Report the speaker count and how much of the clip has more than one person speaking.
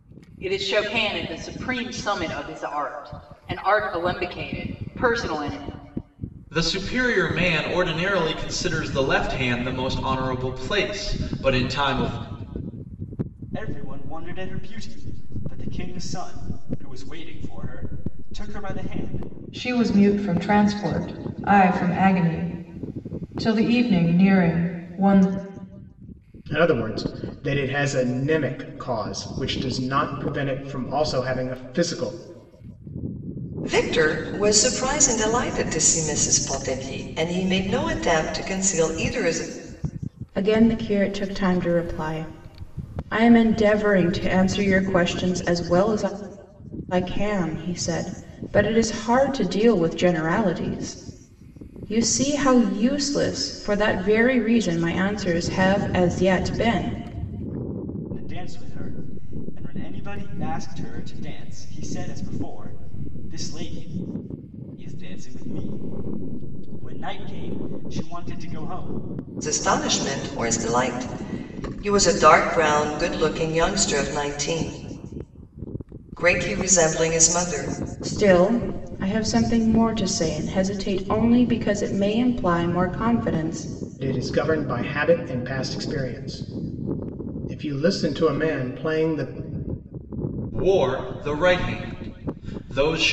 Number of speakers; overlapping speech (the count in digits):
7, no overlap